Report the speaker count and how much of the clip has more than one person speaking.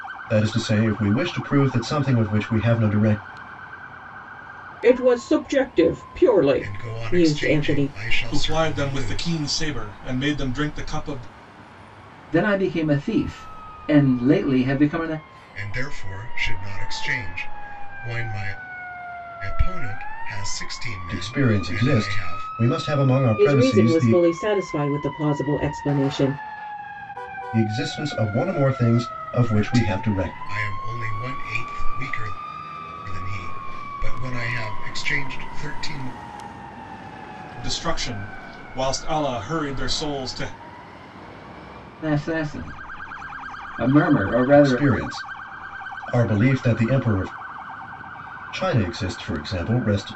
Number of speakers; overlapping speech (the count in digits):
5, about 12%